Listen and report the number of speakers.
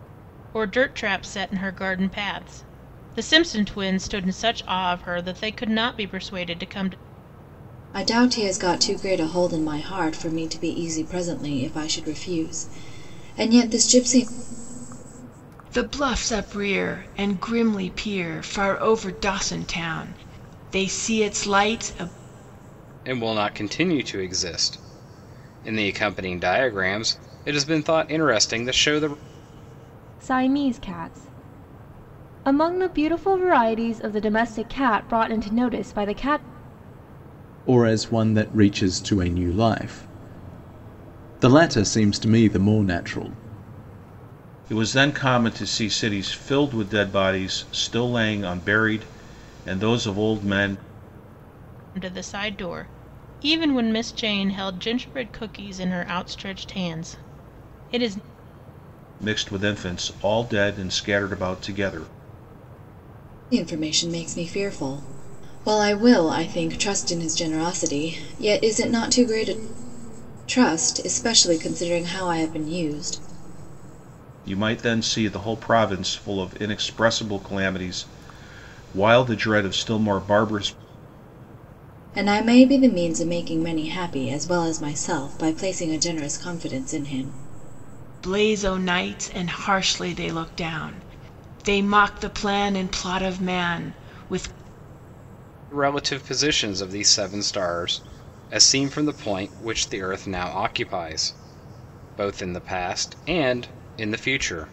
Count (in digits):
7